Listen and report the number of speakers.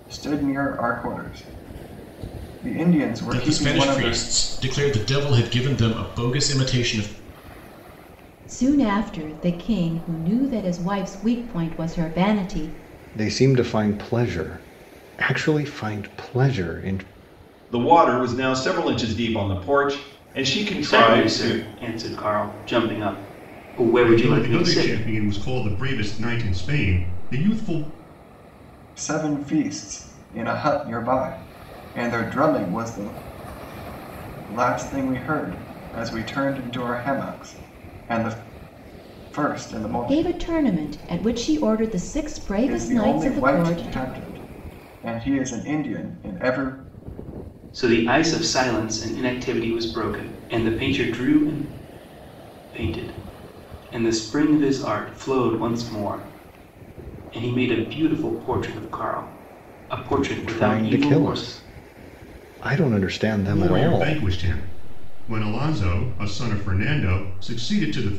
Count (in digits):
7